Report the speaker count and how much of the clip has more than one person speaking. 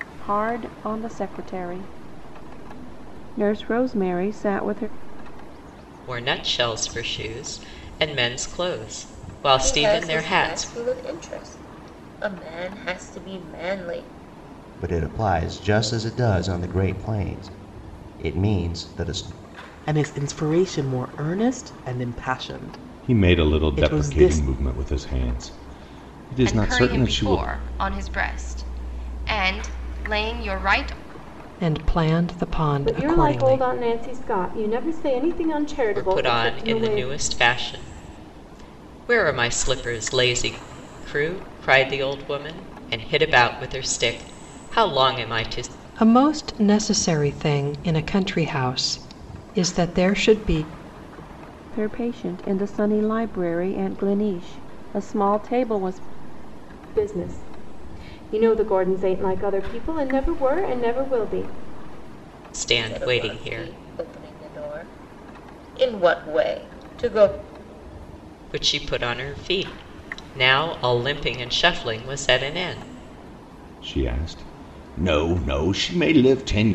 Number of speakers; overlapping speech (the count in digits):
9, about 9%